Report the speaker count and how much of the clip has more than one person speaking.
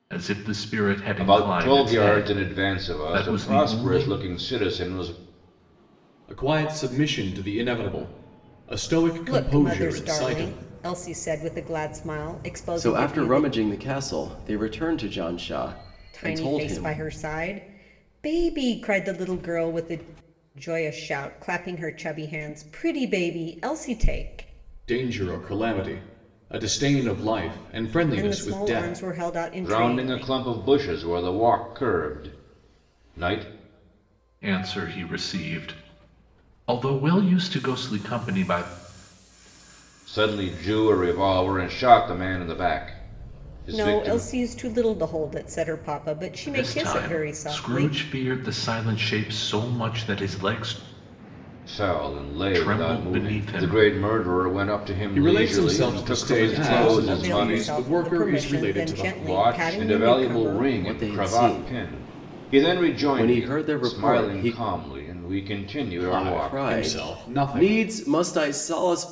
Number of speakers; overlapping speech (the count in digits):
5, about 31%